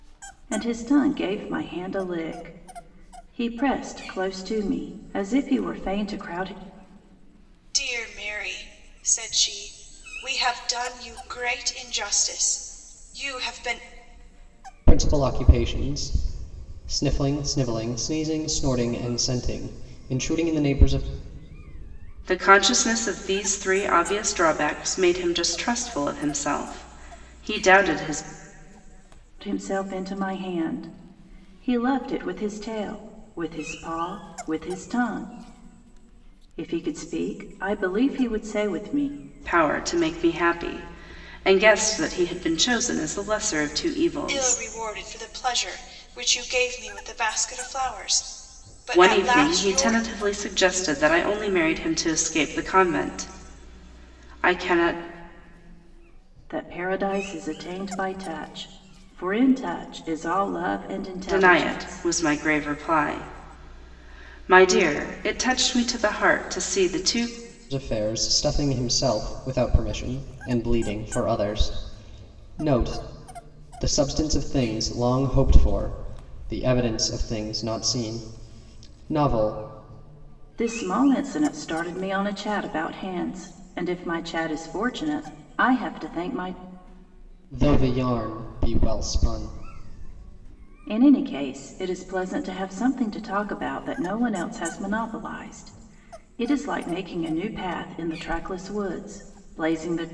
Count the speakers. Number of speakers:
4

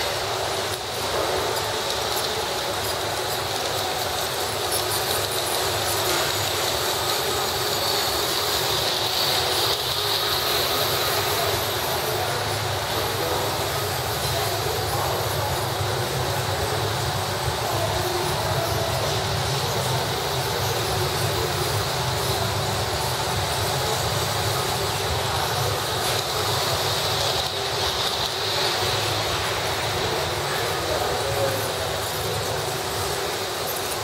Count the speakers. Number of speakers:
0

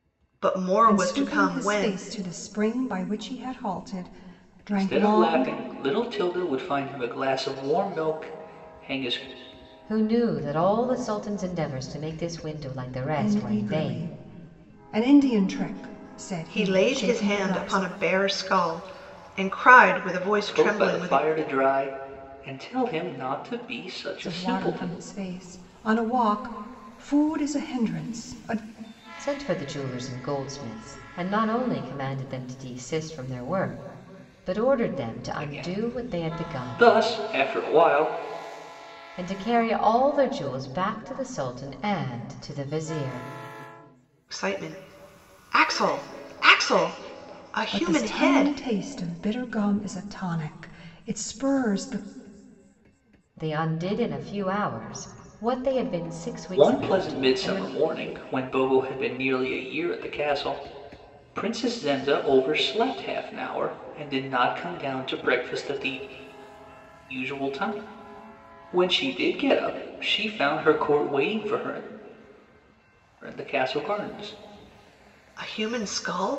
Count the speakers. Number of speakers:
4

